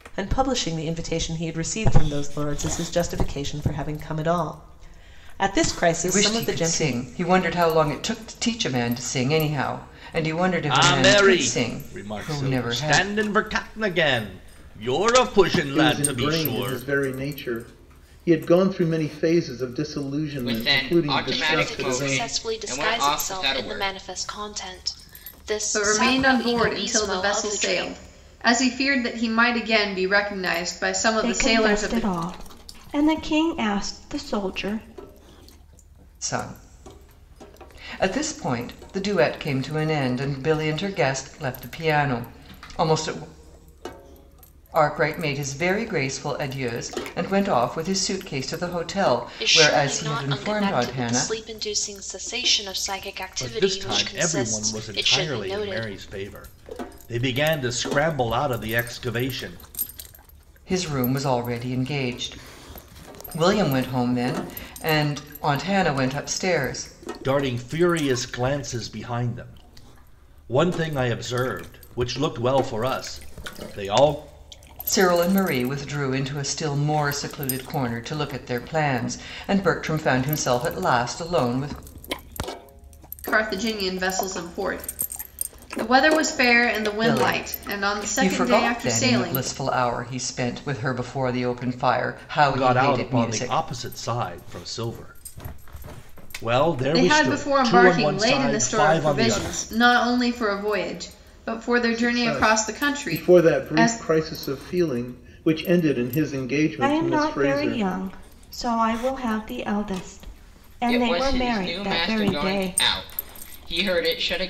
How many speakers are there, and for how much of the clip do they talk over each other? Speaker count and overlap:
8, about 24%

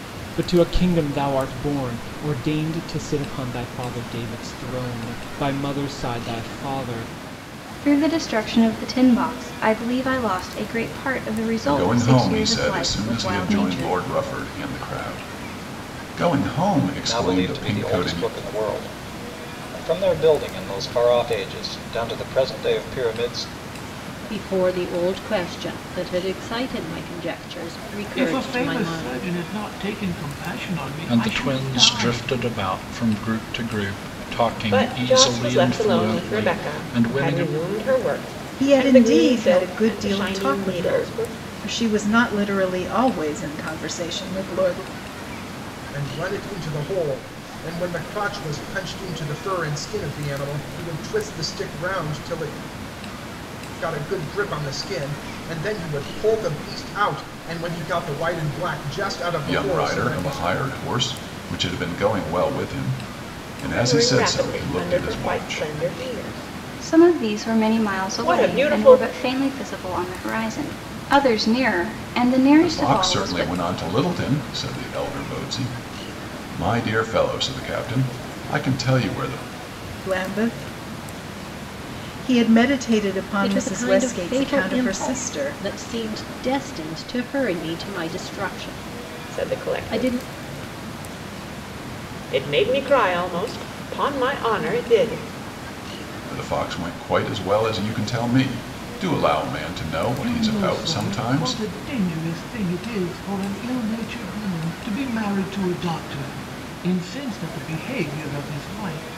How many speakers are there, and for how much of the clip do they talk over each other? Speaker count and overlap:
10, about 21%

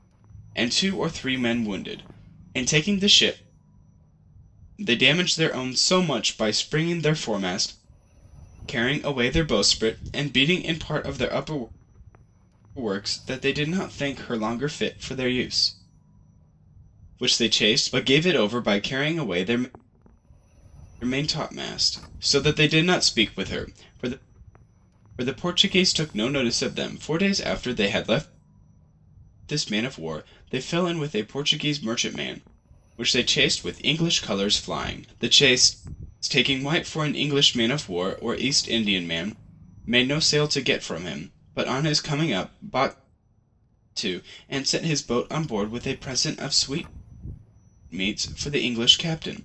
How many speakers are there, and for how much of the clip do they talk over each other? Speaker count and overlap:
1, no overlap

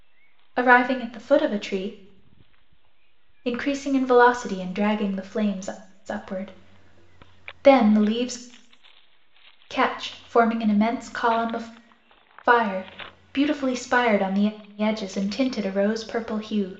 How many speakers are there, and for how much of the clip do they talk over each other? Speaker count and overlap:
1, no overlap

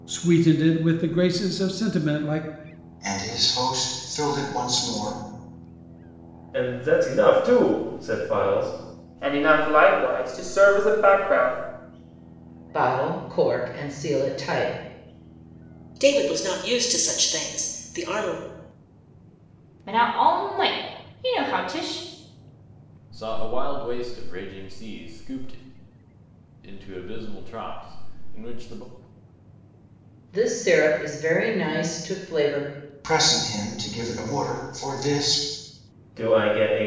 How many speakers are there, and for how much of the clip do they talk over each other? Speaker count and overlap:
8, no overlap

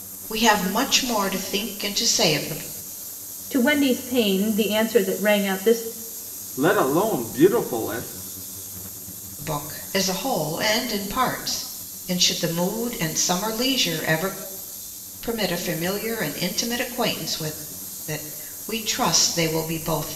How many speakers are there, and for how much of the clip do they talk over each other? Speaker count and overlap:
3, no overlap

